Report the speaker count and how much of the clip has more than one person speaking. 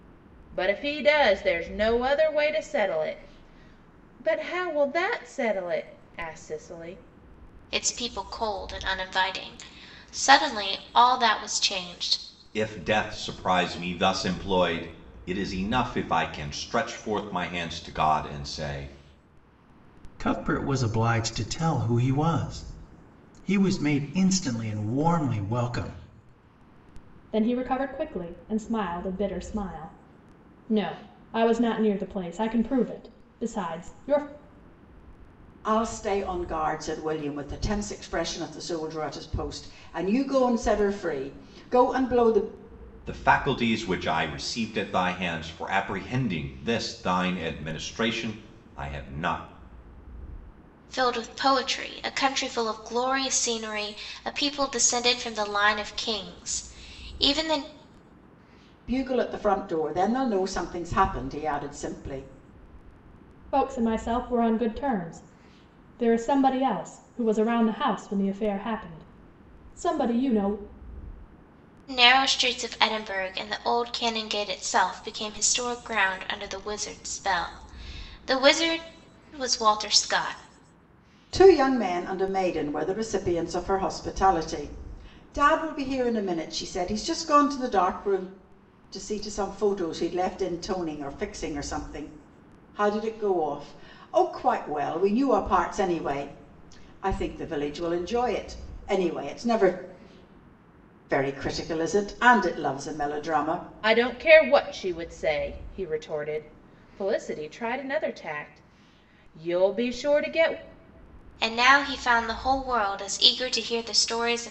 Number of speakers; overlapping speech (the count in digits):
6, no overlap